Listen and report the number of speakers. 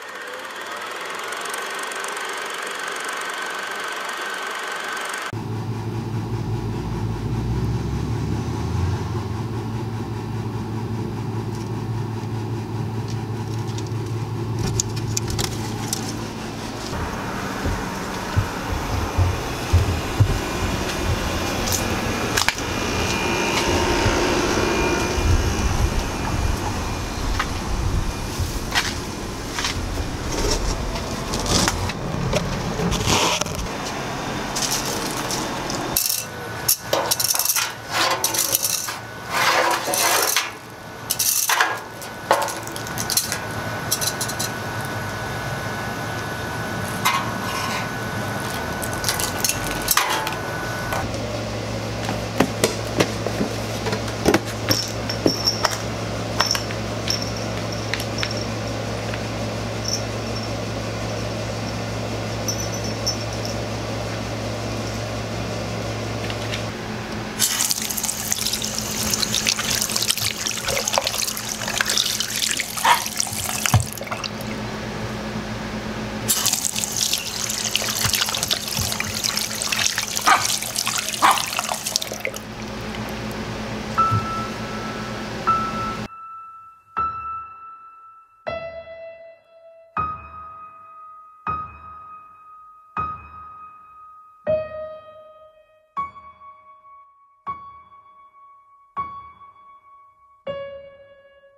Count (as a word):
zero